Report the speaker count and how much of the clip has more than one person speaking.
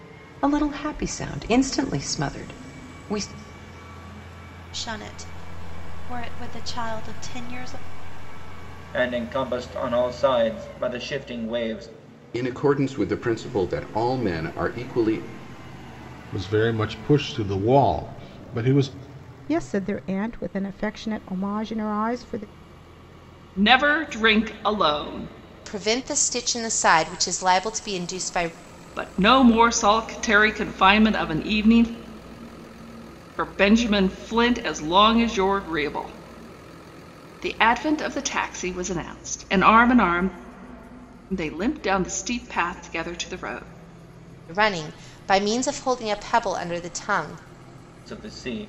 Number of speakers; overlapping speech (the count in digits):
8, no overlap